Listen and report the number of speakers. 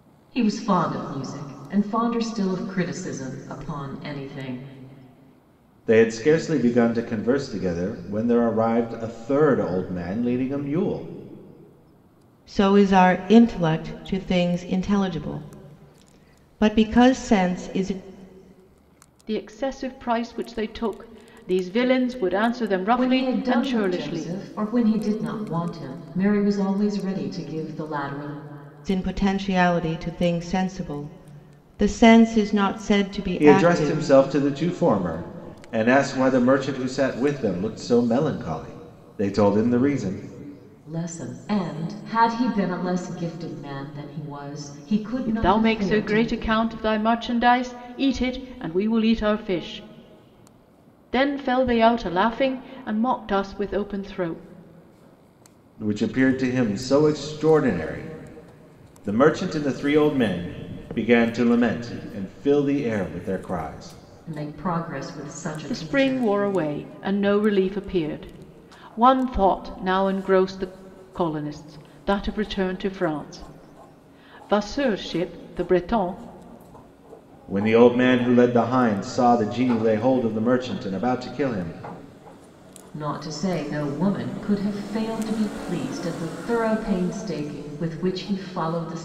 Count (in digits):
4